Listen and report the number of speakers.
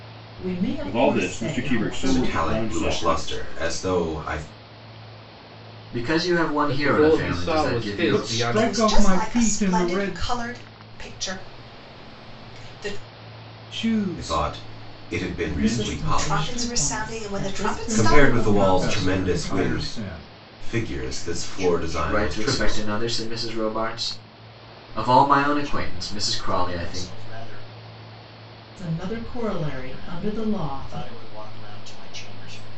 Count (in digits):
8